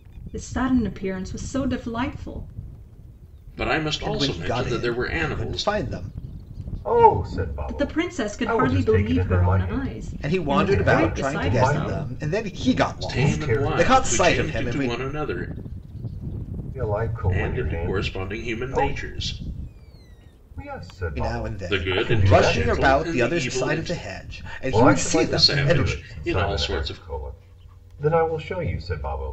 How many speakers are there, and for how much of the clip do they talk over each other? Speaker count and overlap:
4, about 55%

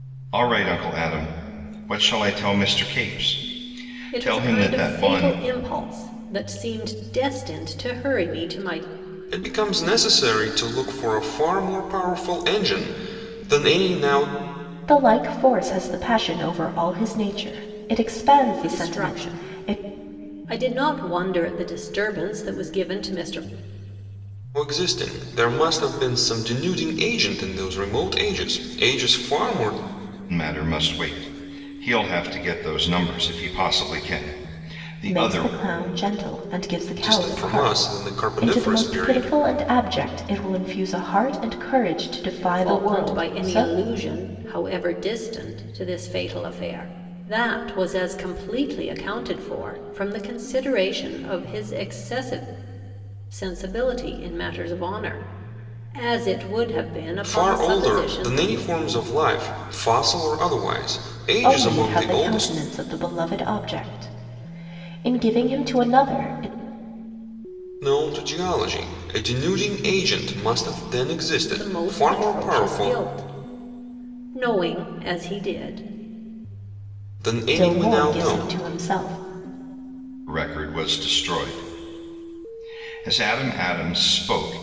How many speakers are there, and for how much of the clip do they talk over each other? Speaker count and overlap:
4, about 13%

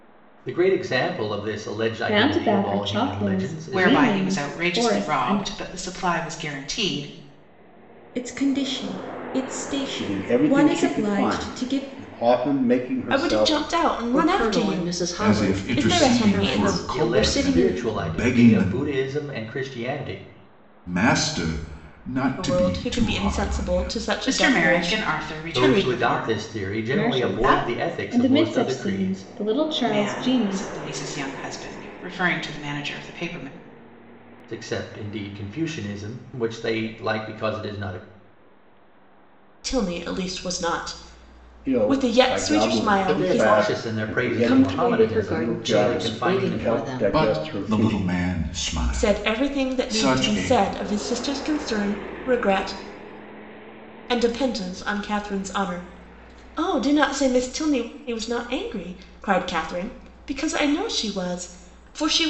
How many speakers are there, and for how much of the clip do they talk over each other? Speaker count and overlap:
8, about 43%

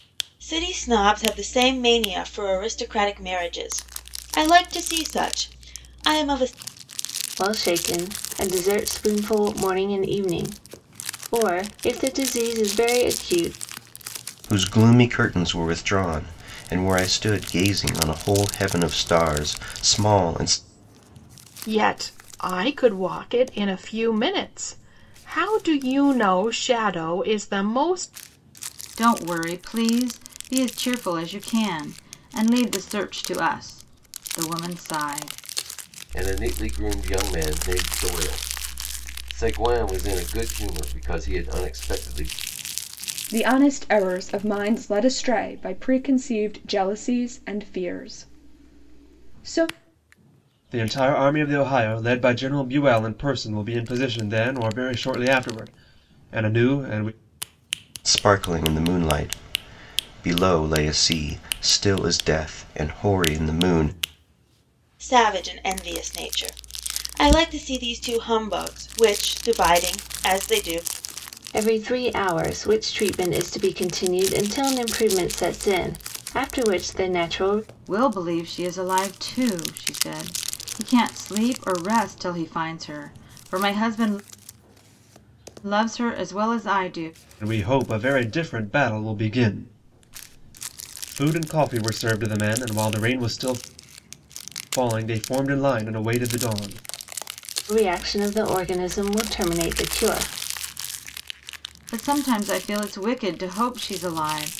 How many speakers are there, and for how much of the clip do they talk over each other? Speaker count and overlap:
8, no overlap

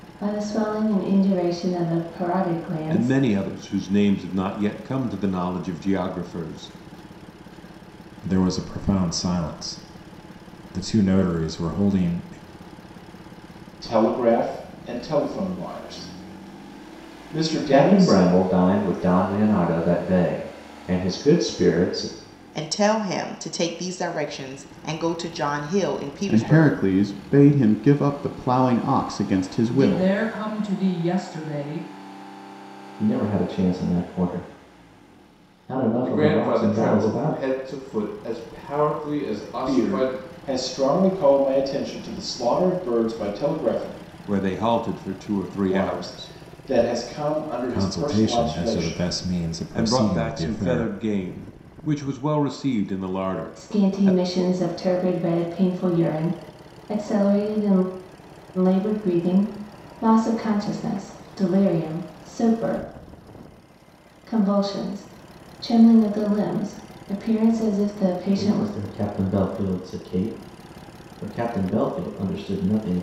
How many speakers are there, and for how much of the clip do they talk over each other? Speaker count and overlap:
10, about 12%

